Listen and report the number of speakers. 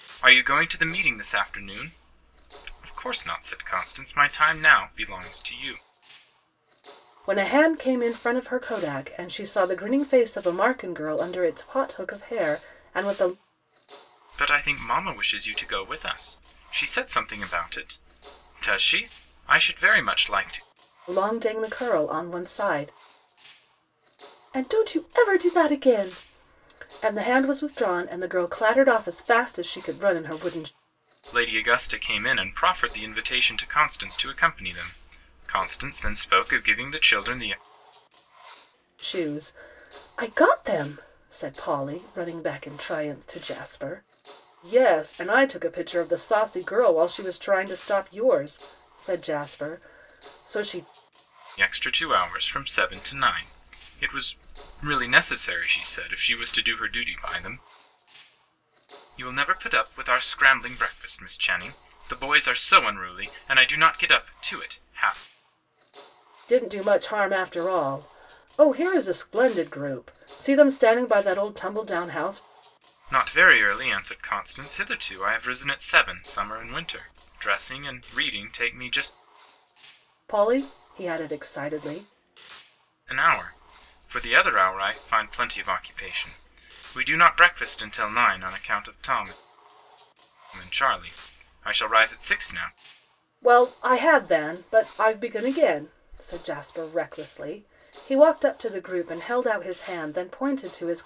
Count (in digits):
2